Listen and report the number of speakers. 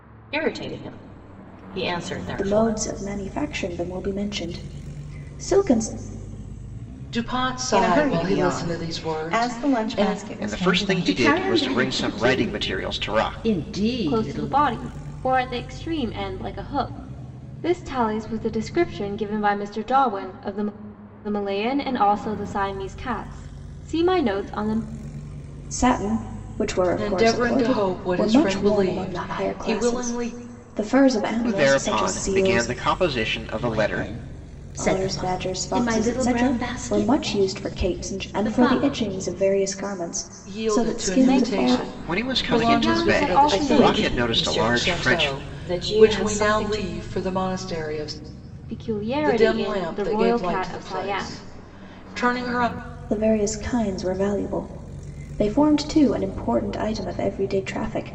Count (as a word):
seven